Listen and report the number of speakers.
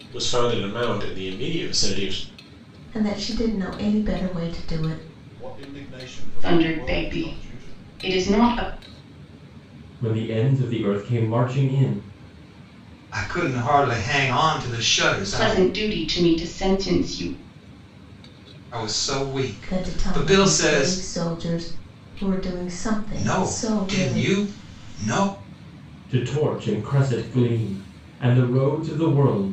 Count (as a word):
six